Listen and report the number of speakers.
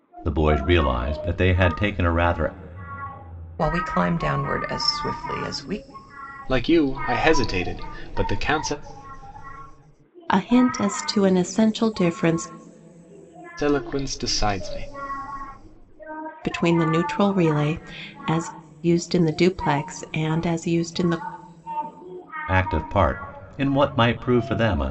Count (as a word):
four